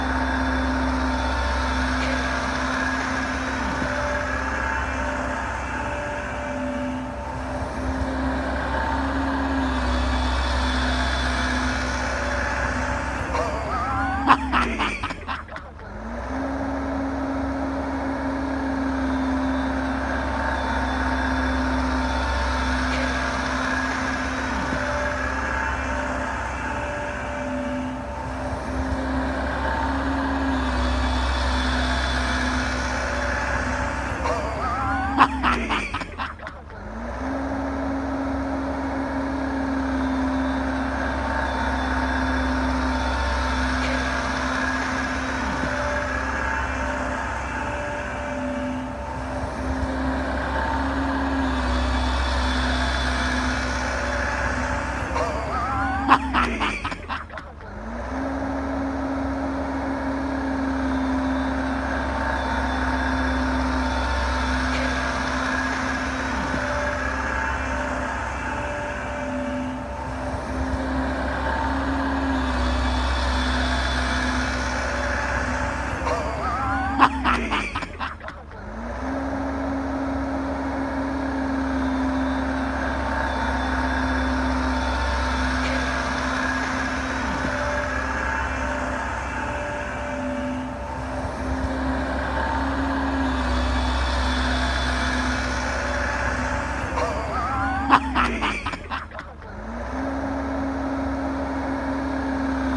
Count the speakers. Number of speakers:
zero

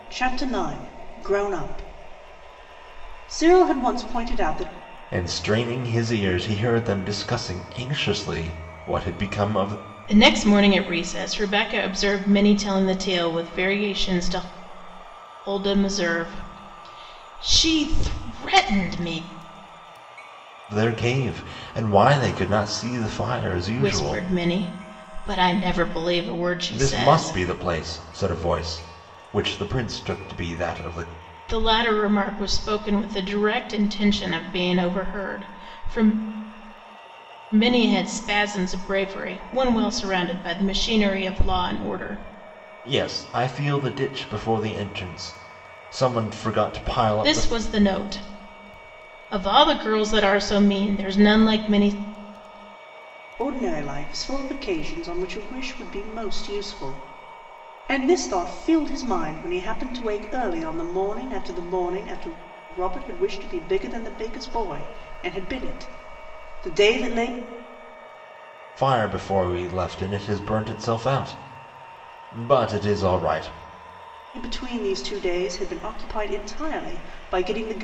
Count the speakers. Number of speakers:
three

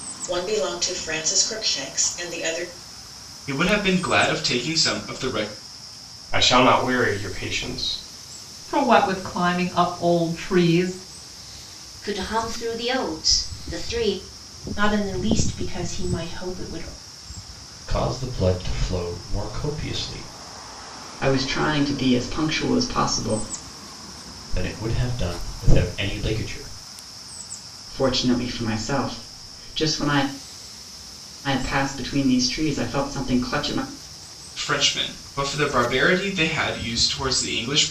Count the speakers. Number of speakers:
eight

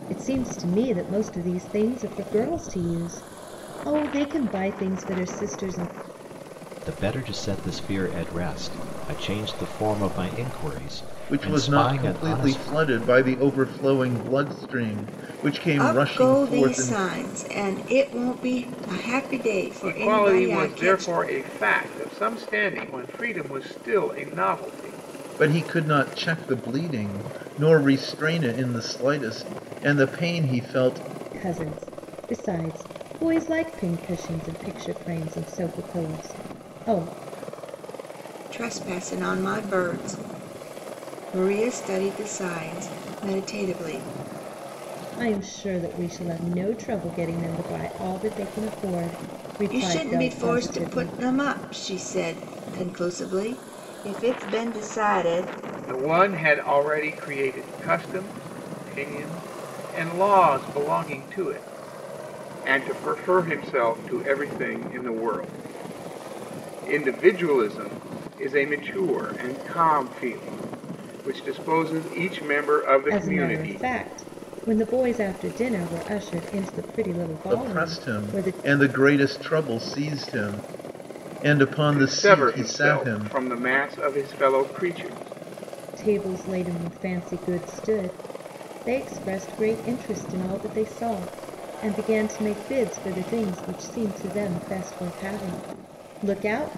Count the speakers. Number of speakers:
five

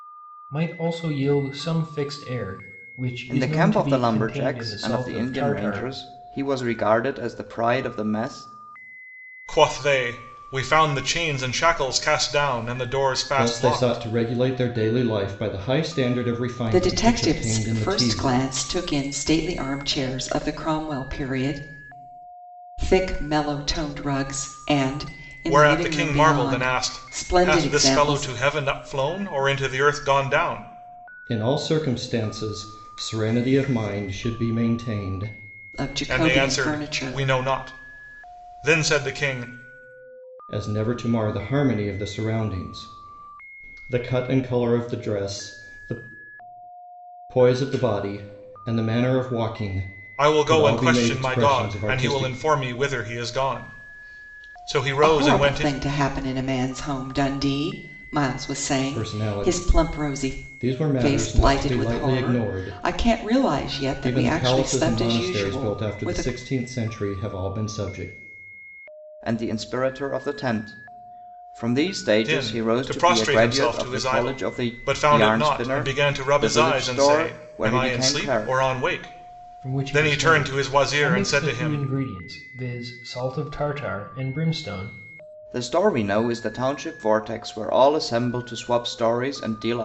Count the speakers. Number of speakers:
five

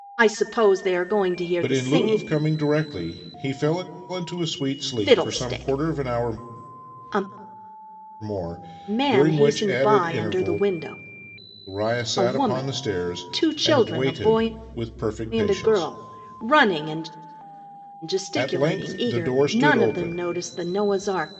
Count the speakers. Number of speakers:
two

